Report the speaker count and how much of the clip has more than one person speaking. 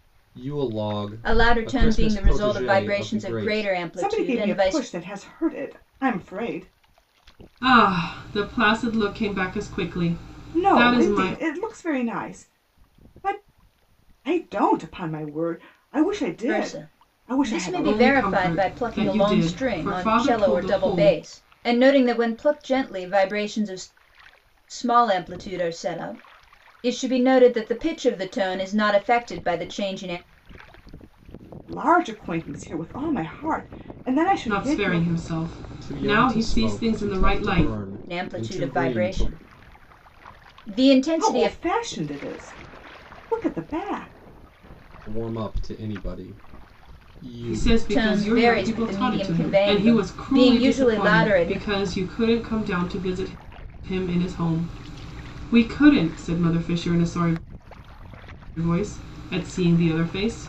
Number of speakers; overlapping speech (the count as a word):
four, about 29%